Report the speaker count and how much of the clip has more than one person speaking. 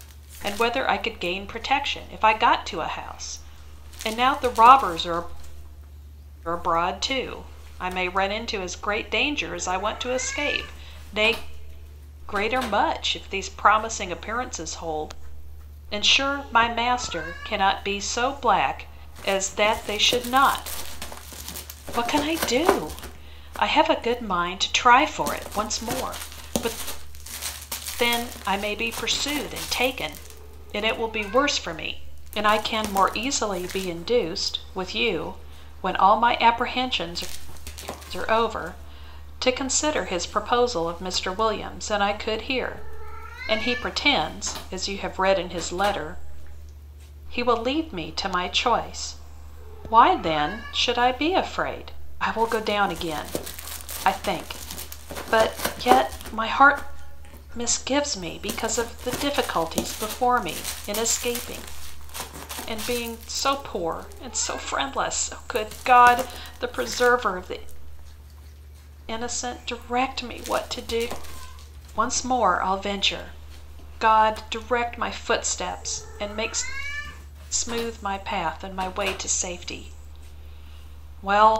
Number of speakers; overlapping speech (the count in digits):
1, no overlap